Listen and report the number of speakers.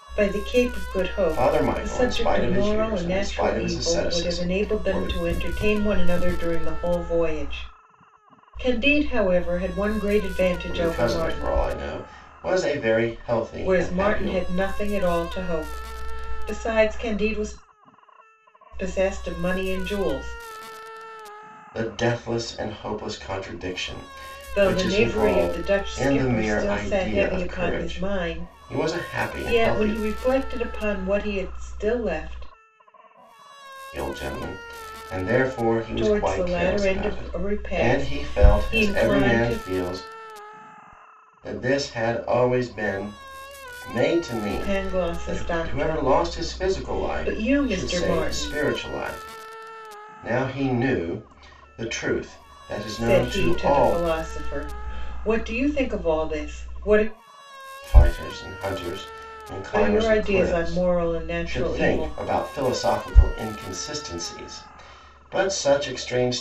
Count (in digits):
2